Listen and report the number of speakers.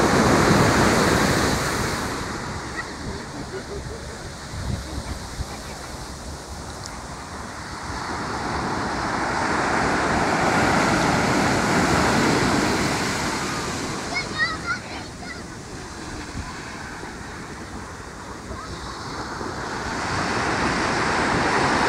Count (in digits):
0